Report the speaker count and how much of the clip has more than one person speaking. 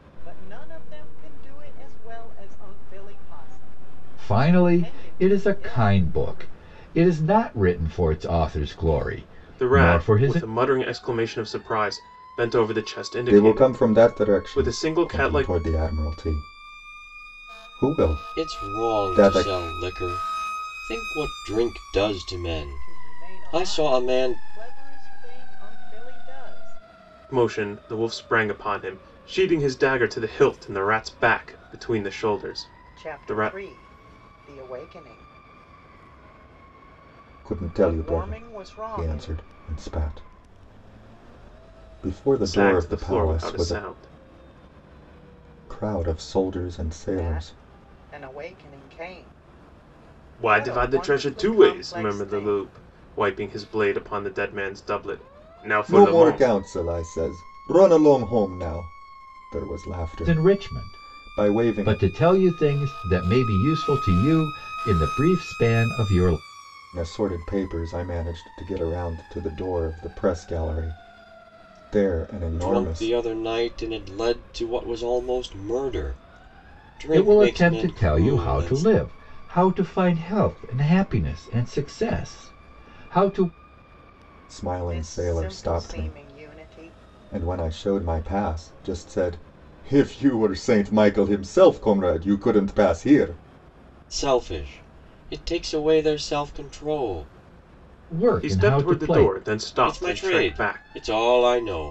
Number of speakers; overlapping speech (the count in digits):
5, about 23%